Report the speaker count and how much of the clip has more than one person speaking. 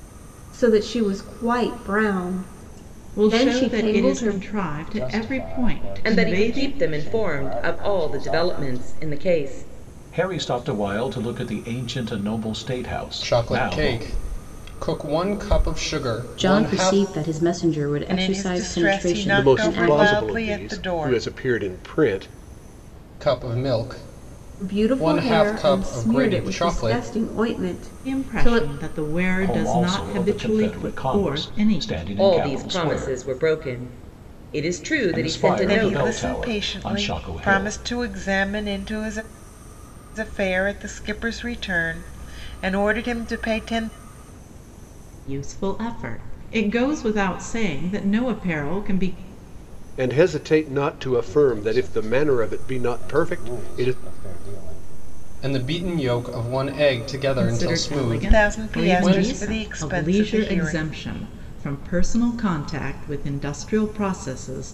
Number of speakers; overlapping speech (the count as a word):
nine, about 40%